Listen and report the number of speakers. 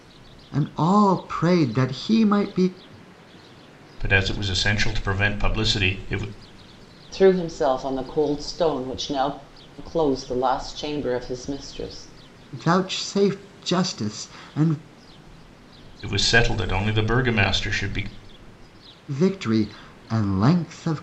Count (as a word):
three